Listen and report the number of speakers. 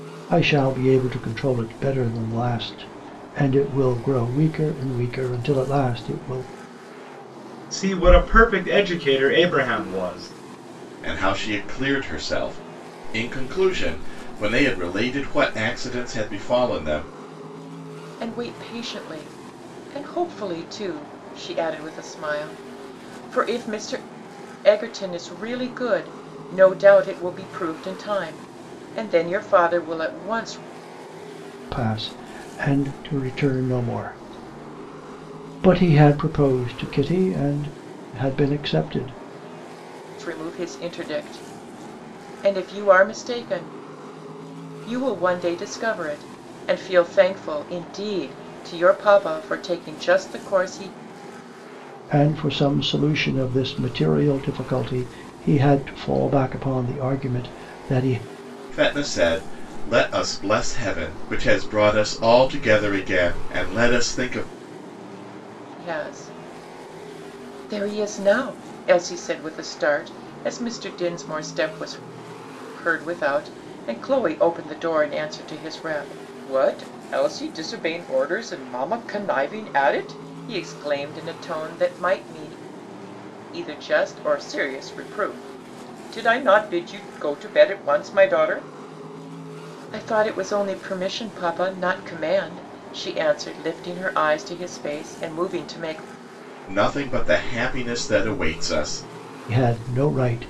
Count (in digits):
4